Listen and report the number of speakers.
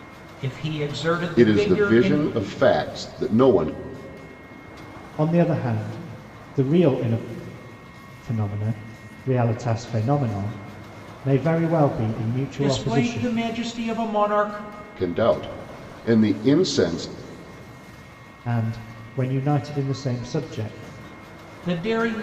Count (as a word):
three